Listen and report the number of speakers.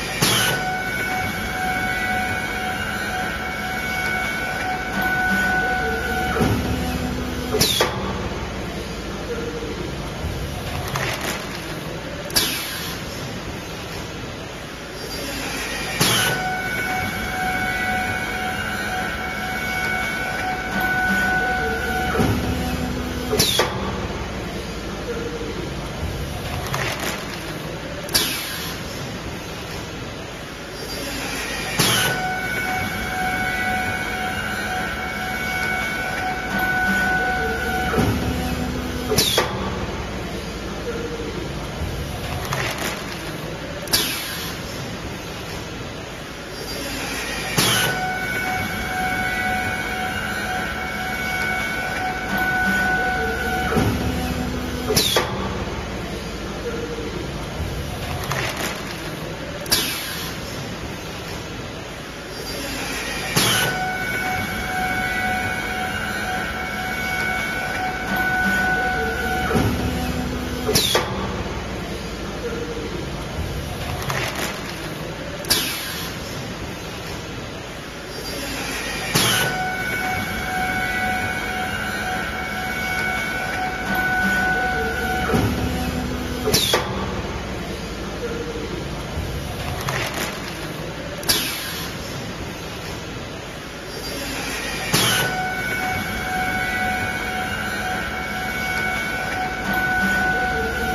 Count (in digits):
0